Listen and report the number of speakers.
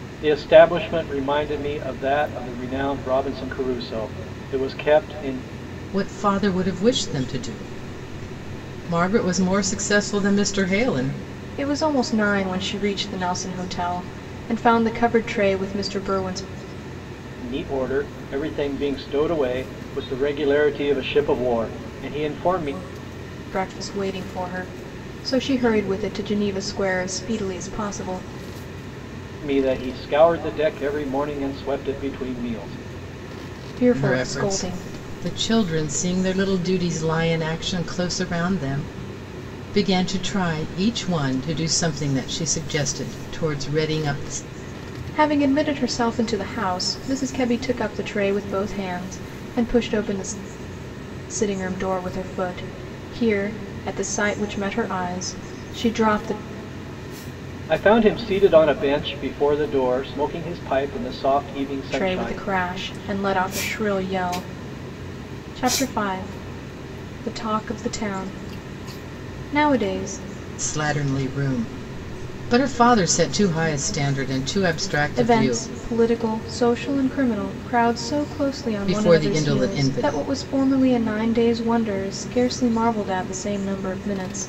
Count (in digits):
3